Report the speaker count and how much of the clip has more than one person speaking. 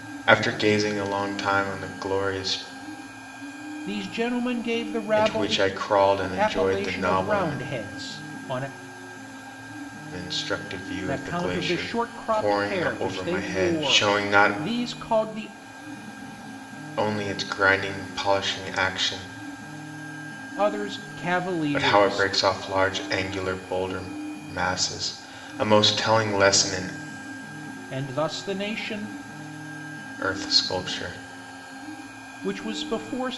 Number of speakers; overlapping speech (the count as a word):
two, about 17%